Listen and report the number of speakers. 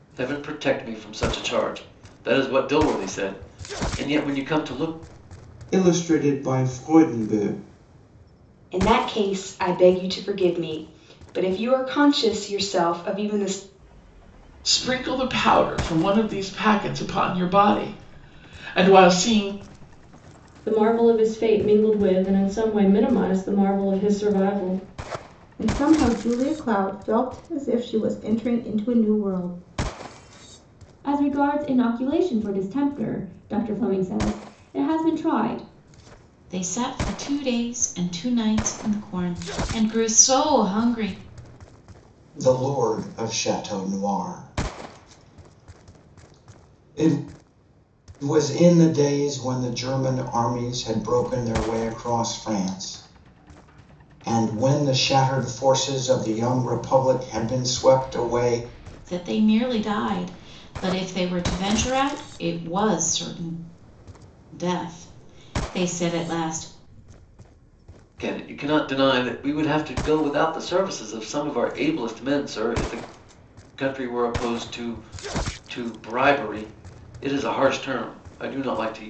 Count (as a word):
eight